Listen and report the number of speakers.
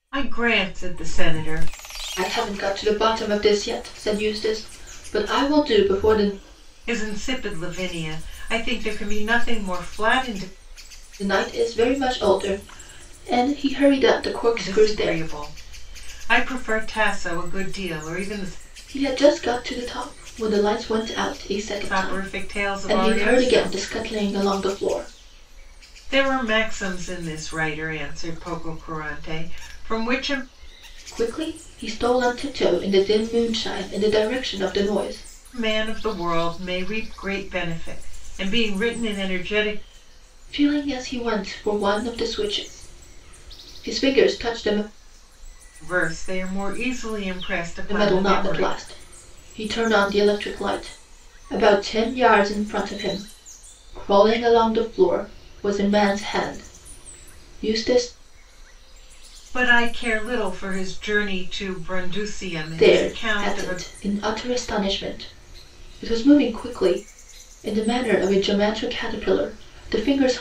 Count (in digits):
2